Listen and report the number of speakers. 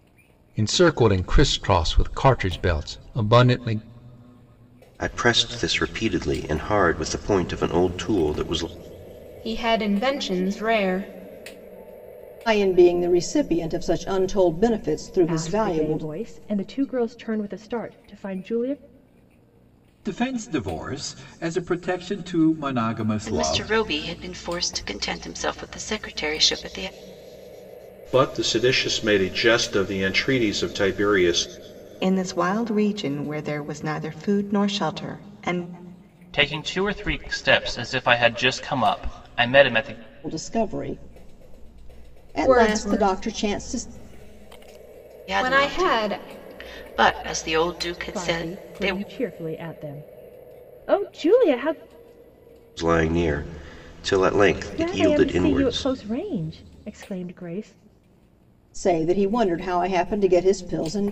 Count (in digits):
10